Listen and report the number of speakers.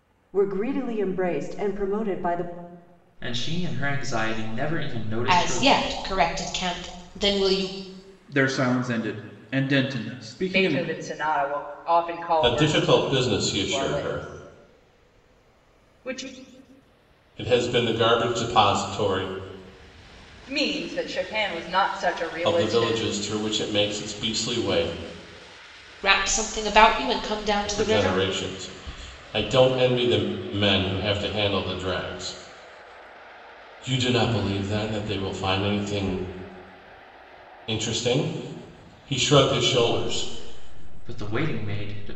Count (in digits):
6